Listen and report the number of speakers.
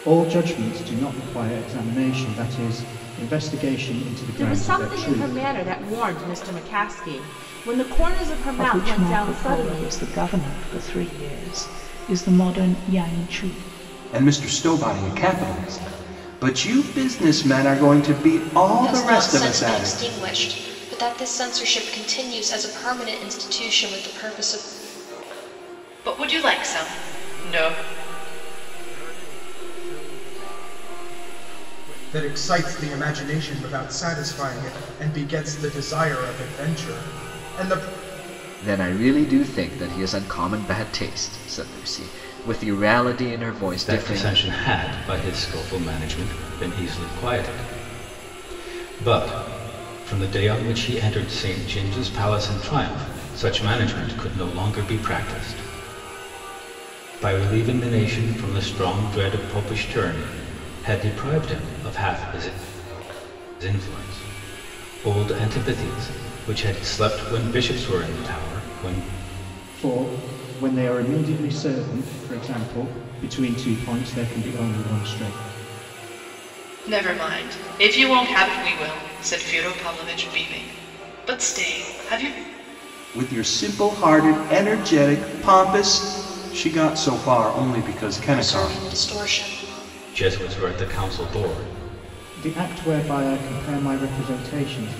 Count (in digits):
10